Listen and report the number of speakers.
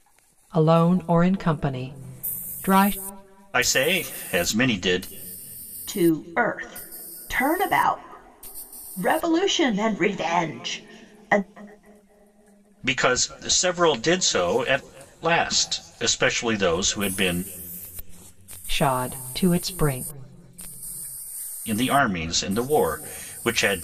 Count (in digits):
3